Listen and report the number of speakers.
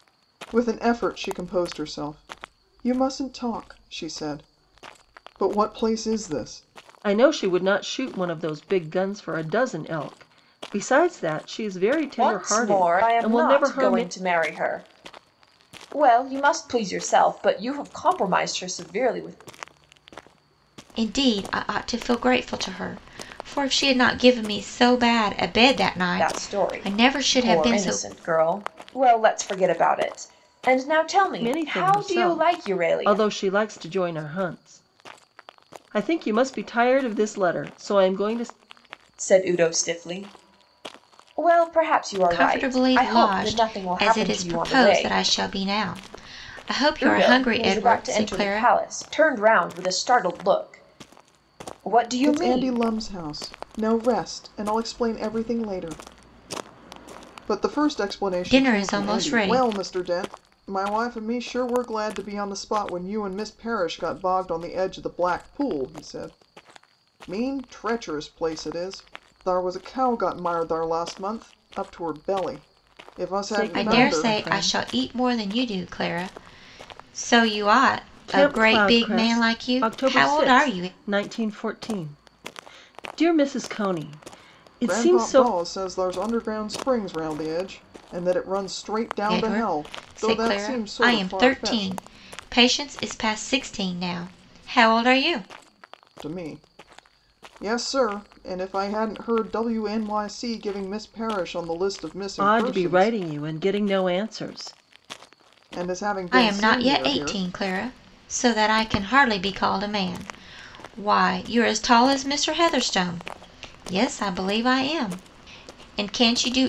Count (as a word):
four